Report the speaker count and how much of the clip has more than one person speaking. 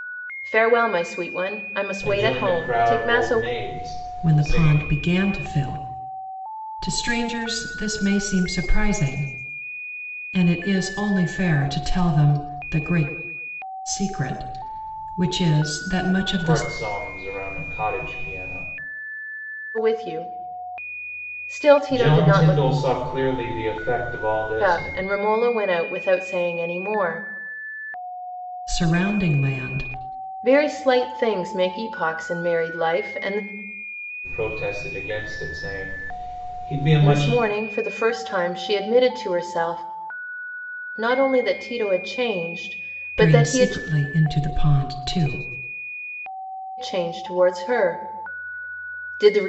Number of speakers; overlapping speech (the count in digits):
3, about 10%